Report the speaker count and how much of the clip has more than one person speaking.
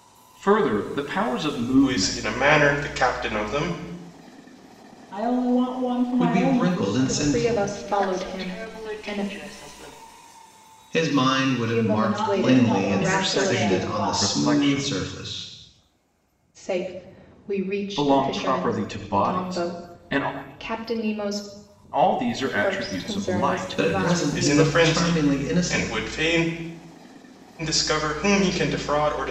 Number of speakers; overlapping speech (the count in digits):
6, about 44%